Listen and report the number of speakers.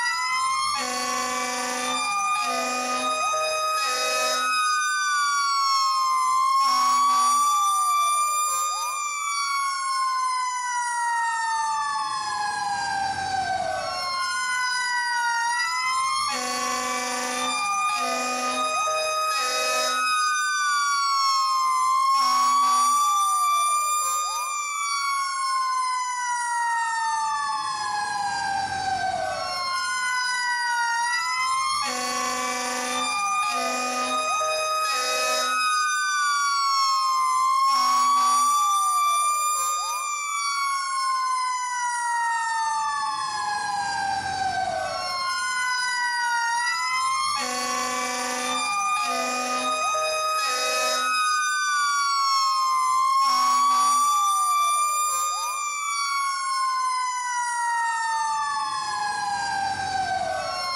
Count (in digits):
0